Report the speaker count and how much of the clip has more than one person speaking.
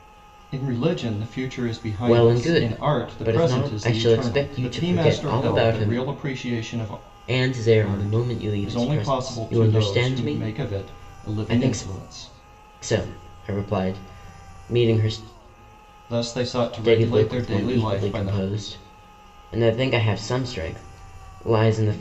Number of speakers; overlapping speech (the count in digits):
2, about 44%